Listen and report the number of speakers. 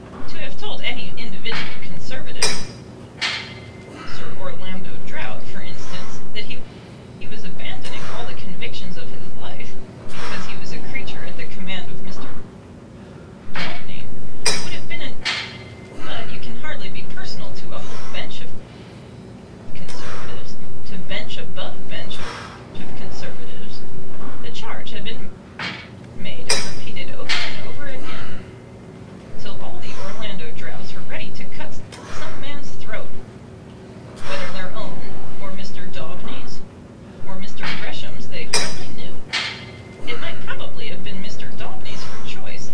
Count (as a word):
one